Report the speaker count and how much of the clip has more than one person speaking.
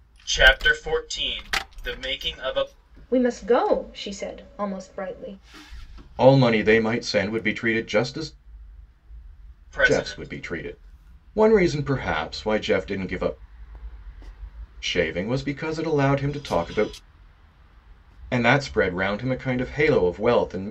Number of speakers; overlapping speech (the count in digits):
3, about 3%